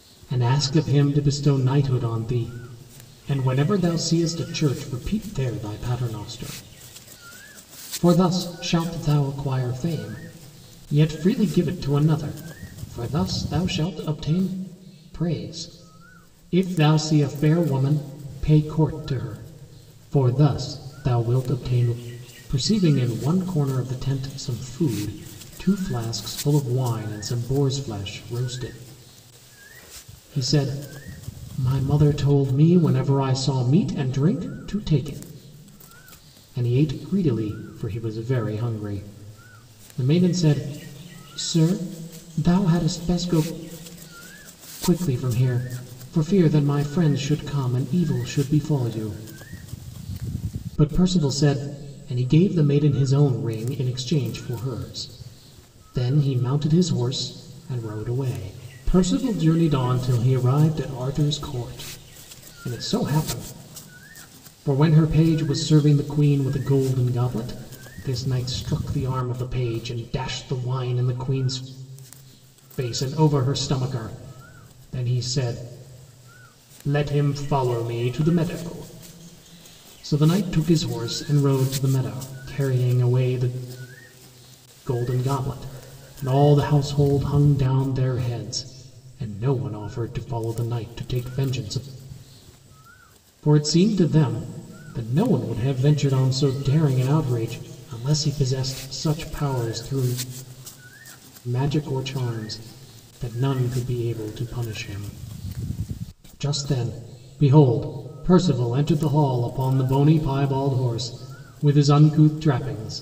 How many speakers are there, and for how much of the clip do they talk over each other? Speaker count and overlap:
one, no overlap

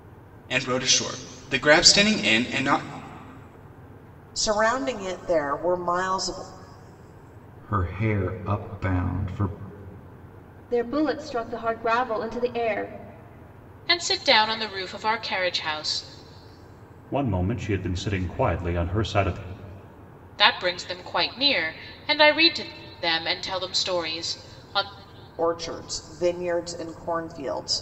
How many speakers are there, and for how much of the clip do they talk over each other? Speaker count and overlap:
six, no overlap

